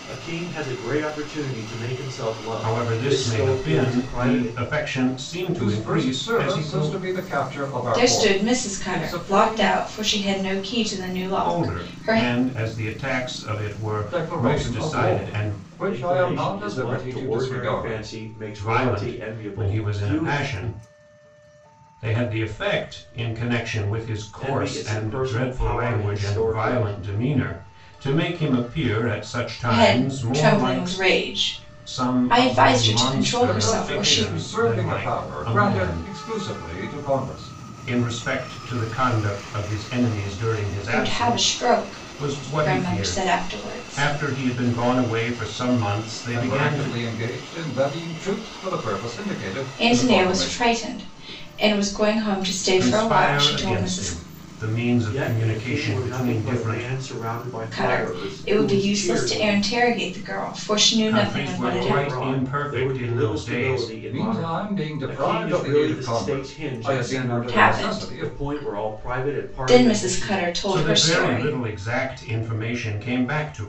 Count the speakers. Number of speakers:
4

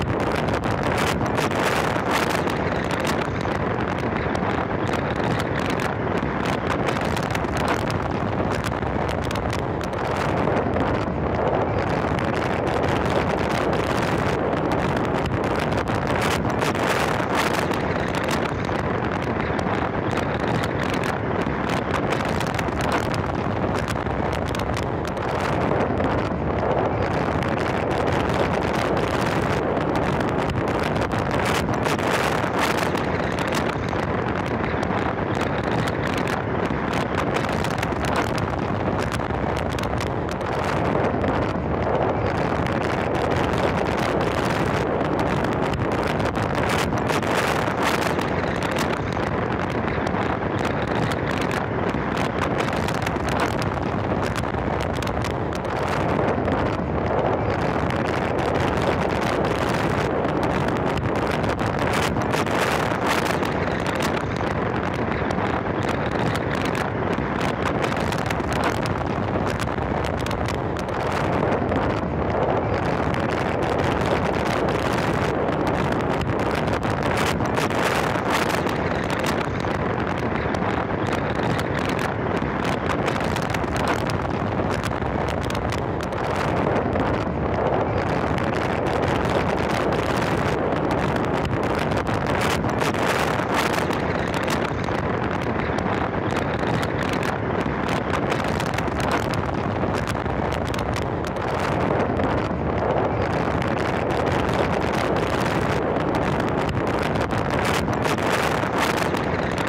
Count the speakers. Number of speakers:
0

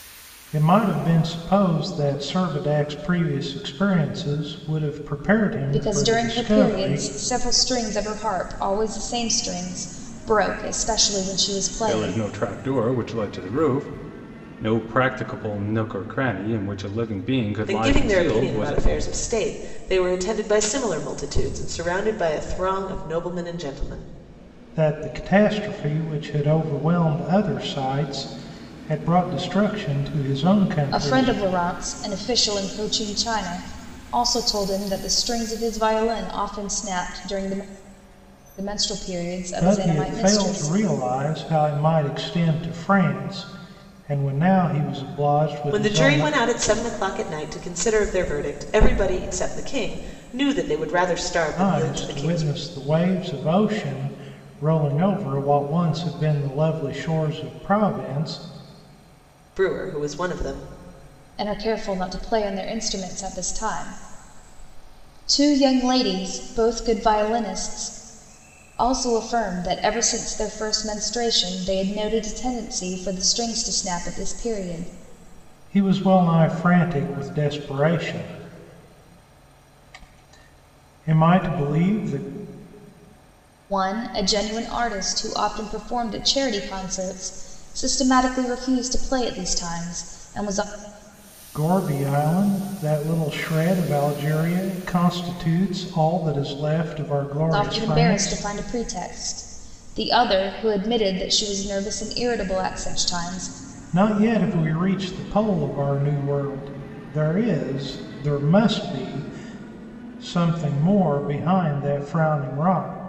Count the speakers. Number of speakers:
4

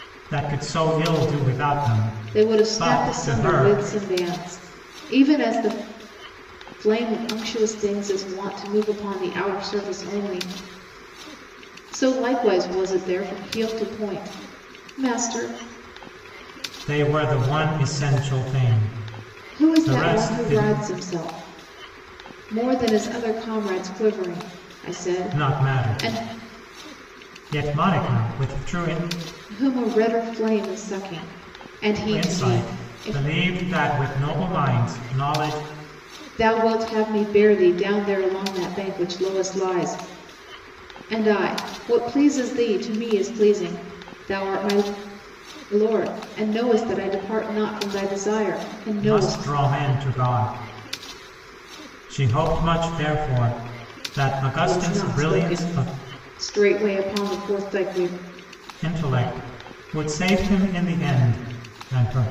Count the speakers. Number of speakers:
2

